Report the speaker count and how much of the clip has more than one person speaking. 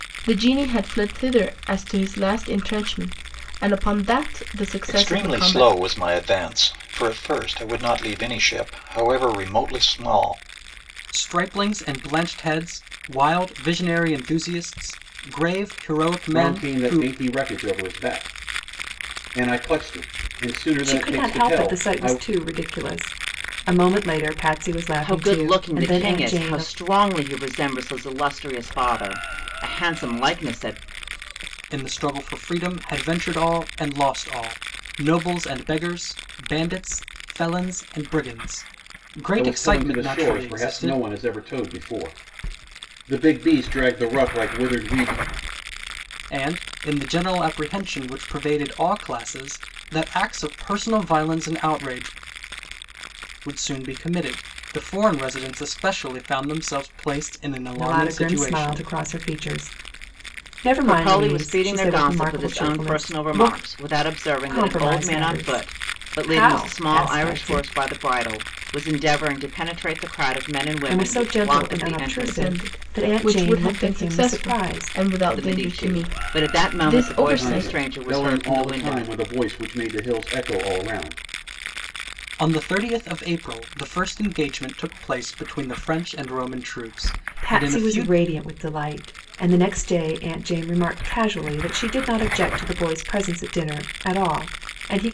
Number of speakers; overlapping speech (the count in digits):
6, about 24%